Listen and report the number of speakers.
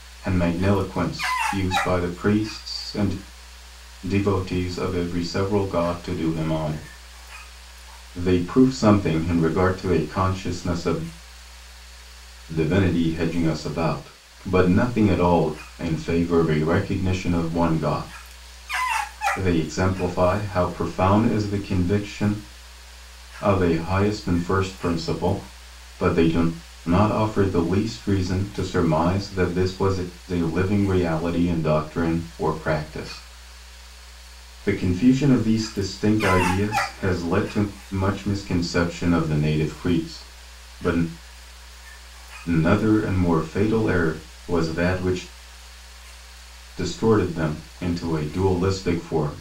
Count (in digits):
1